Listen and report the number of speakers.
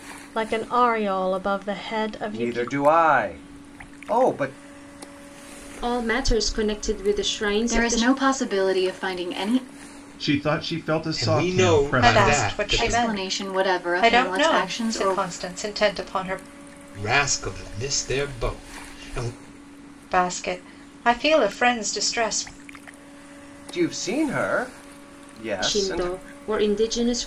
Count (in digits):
7